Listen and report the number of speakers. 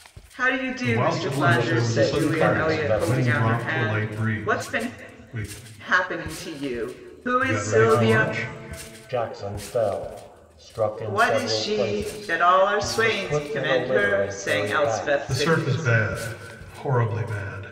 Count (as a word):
three